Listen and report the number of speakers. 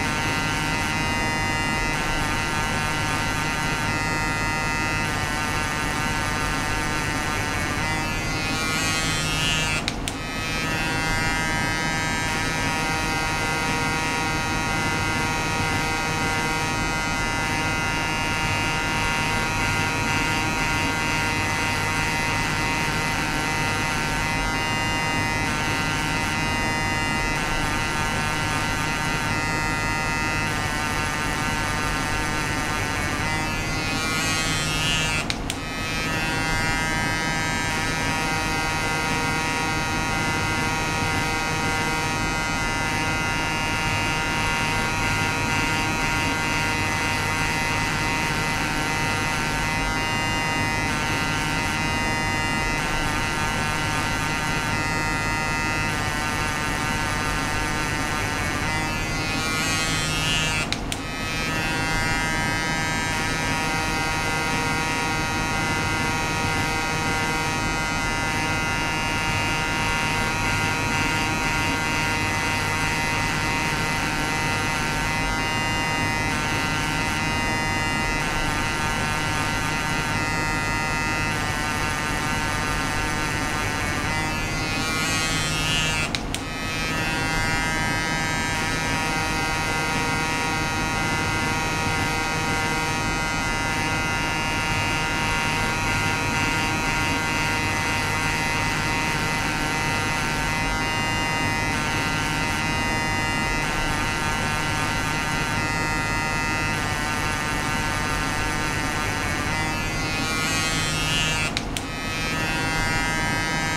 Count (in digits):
0